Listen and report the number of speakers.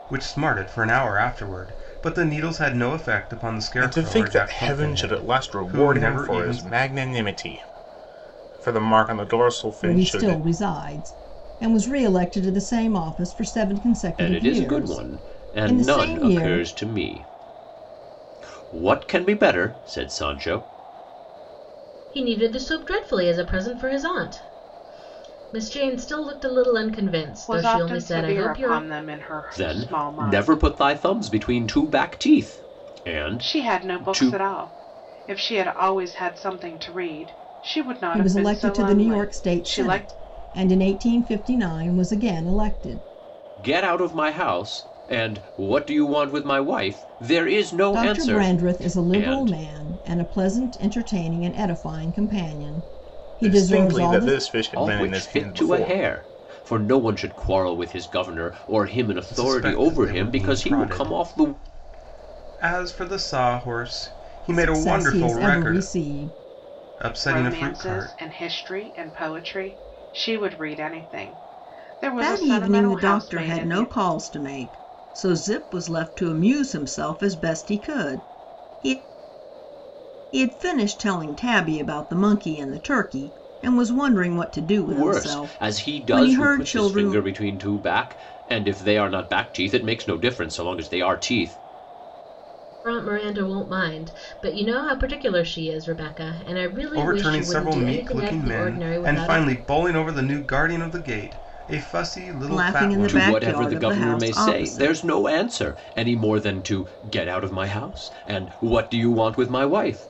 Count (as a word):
six